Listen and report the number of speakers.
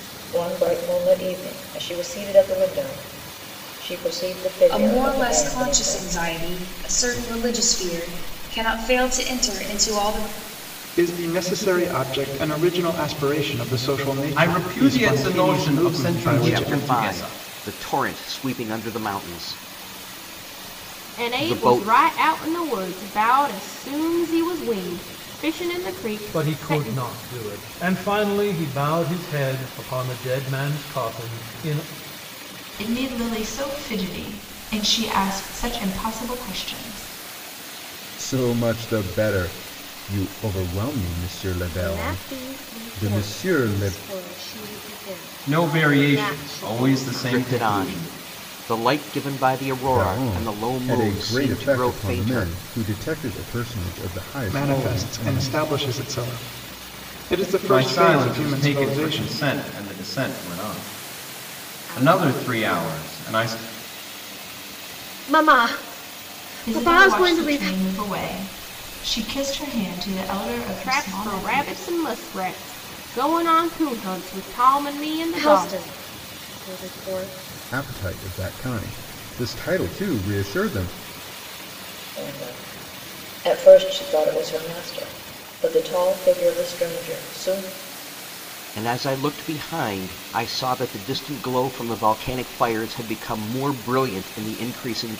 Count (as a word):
ten